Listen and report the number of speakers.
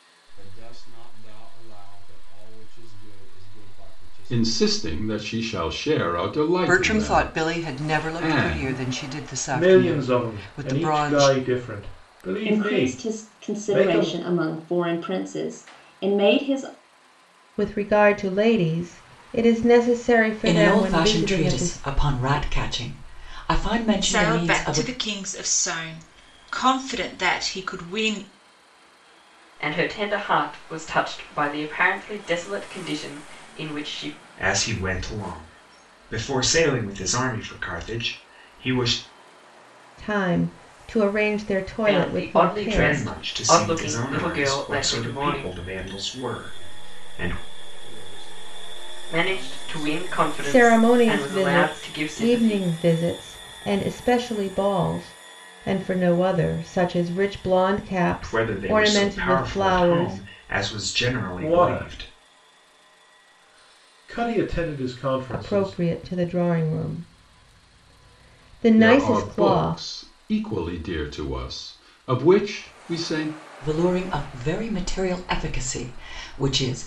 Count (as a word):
ten